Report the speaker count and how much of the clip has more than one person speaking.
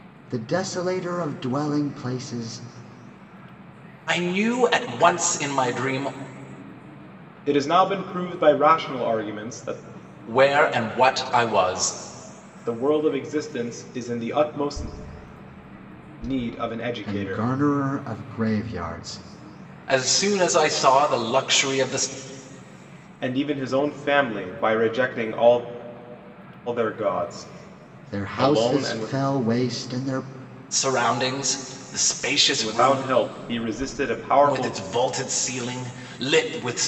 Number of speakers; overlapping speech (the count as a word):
three, about 6%